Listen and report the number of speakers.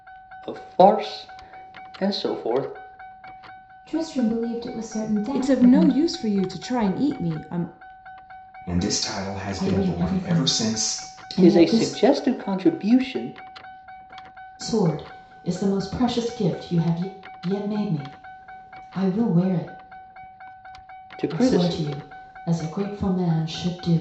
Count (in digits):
5